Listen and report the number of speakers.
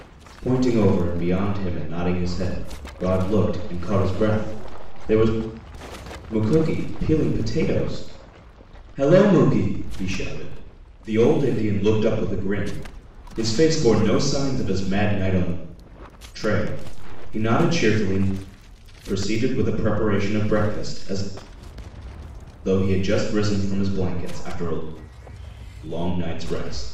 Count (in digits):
1